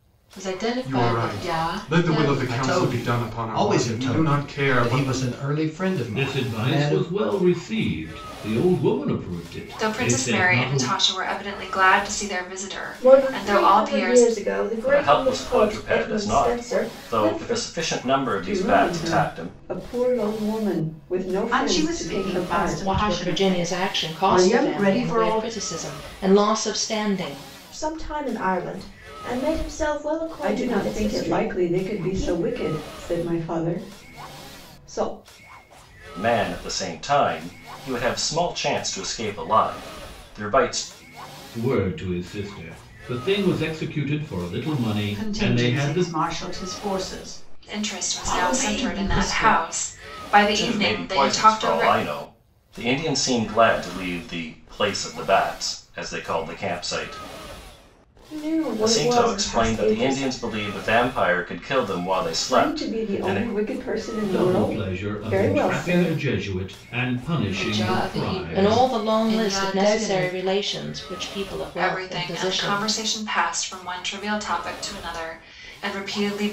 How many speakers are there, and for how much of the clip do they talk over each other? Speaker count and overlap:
ten, about 40%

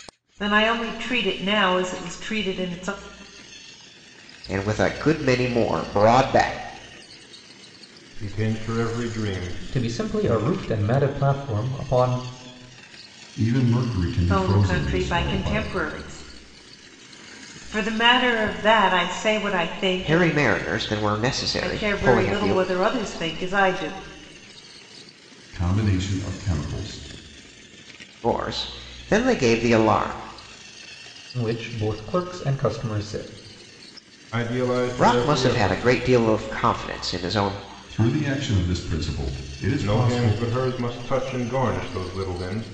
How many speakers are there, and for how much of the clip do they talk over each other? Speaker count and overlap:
five, about 12%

